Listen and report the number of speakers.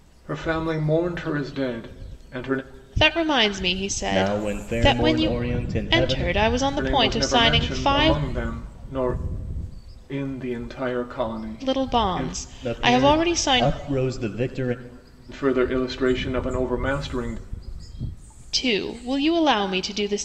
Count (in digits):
3